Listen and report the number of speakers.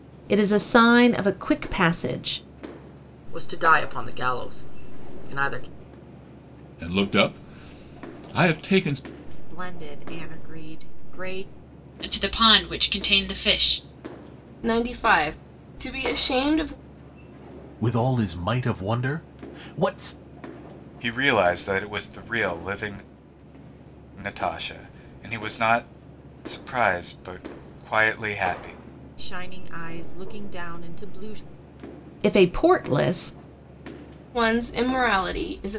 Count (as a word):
eight